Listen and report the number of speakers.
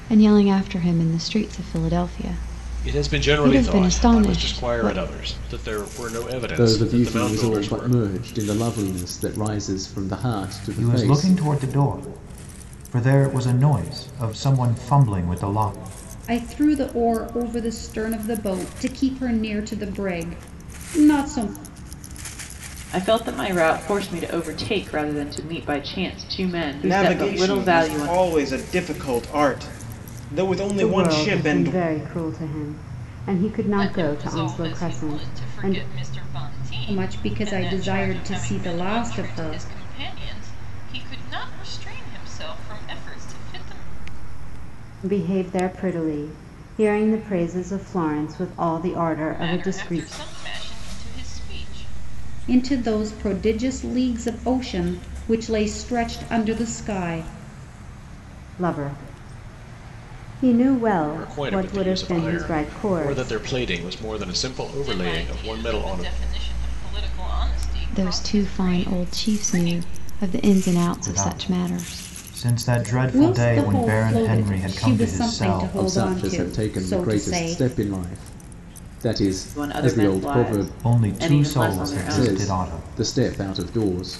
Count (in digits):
9